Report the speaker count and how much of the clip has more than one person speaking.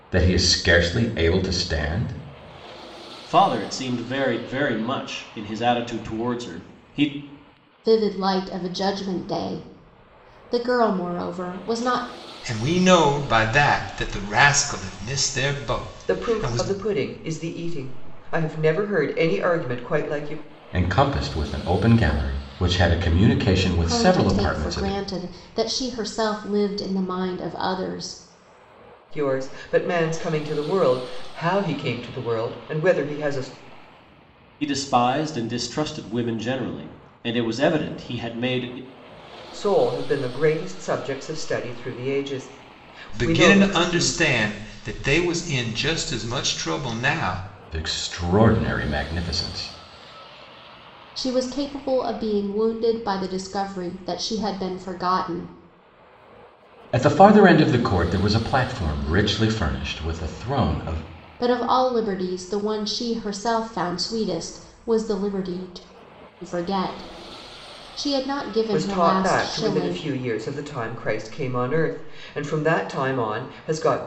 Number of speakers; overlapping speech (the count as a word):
five, about 6%